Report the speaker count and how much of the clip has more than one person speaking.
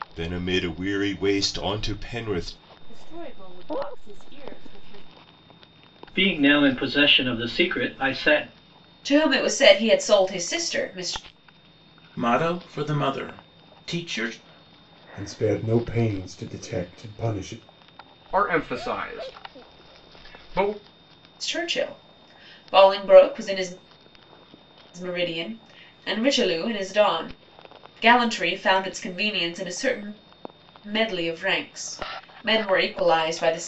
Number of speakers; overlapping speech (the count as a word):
seven, no overlap